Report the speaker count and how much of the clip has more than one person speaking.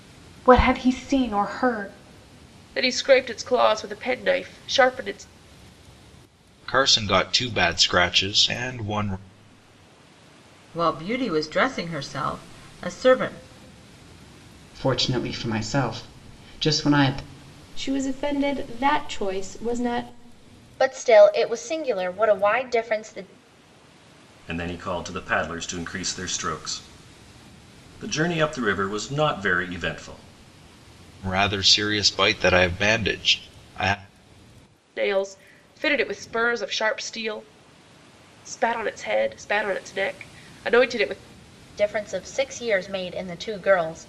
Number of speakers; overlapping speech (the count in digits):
8, no overlap